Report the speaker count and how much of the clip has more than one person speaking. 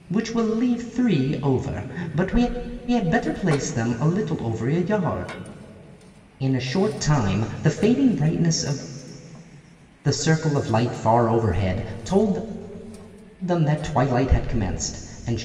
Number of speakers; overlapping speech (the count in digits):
1, no overlap